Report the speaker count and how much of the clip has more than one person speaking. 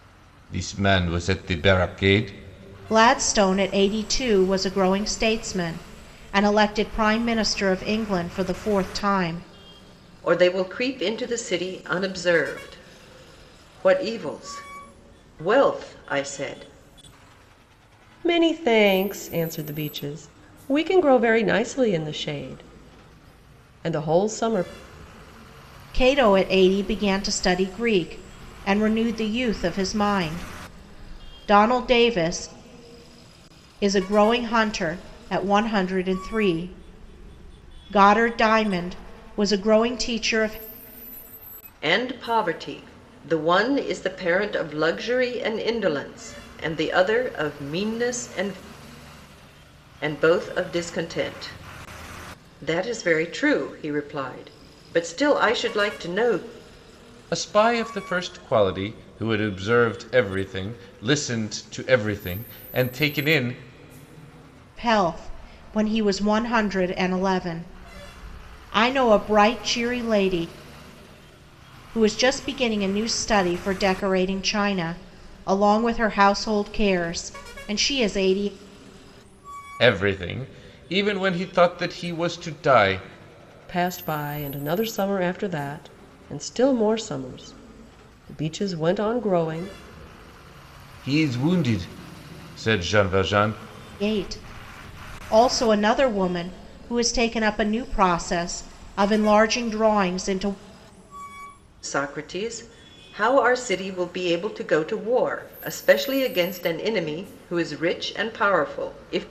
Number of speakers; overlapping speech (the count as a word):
four, no overlap